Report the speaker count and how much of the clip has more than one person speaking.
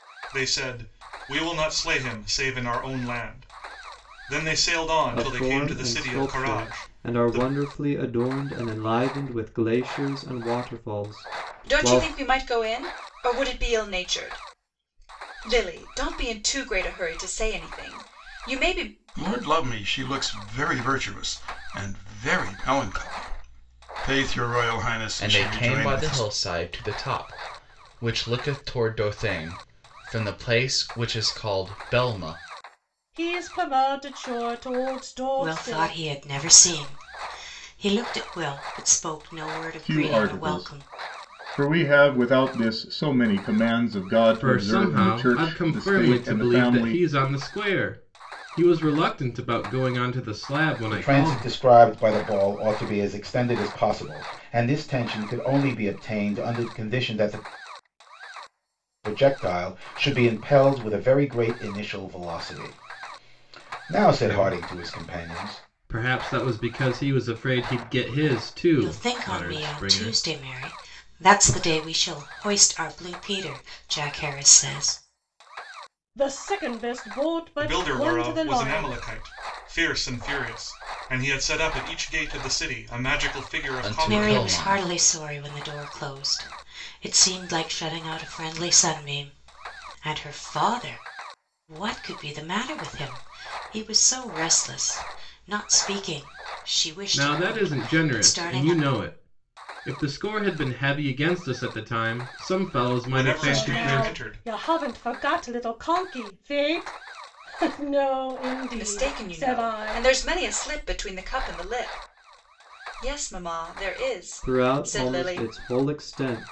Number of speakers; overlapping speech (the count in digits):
10, about 17%